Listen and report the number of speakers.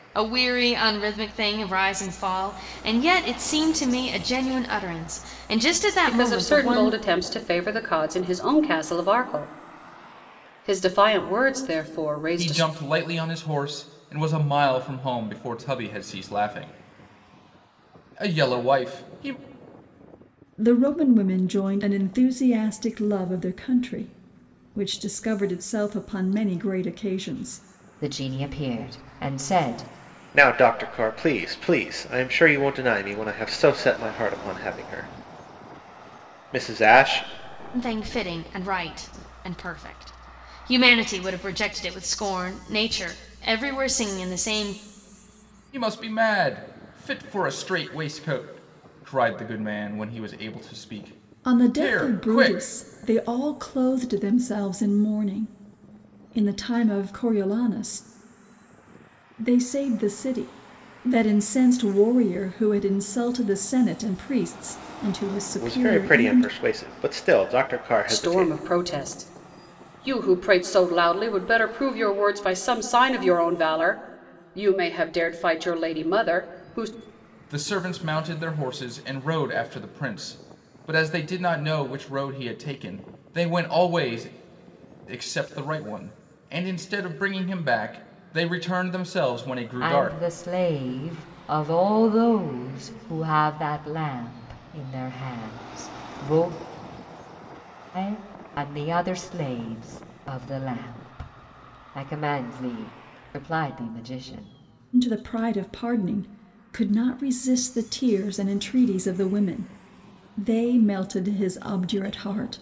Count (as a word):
six